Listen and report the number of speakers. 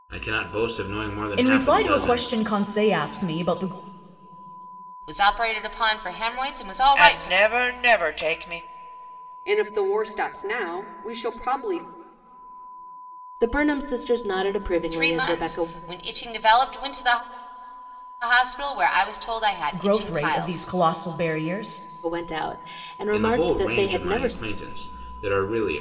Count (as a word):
six